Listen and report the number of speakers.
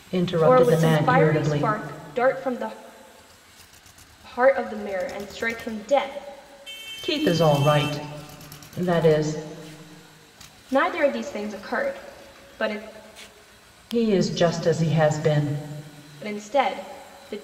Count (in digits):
2